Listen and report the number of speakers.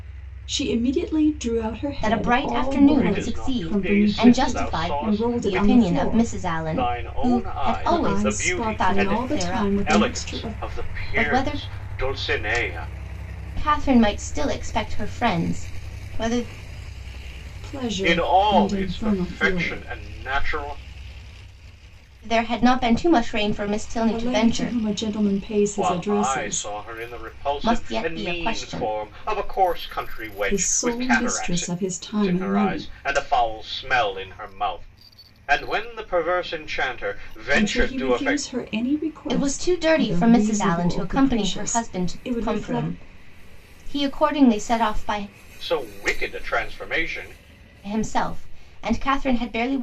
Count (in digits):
3